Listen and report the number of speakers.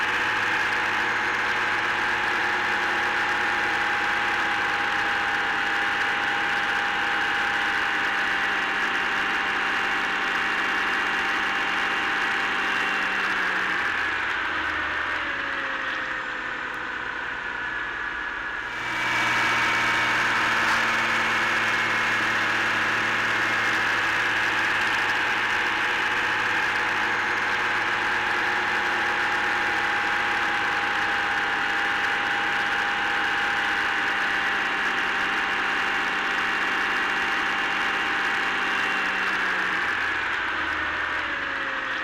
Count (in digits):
0